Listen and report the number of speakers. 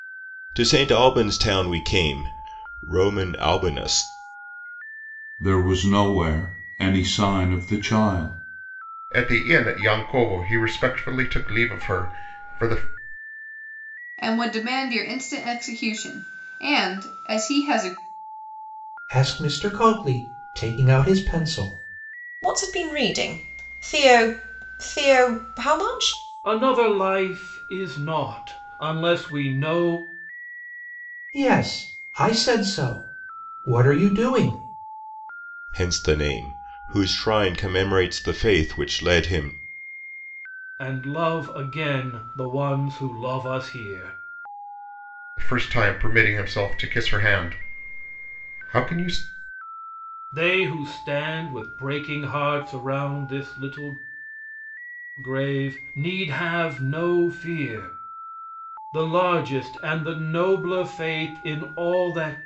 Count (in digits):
7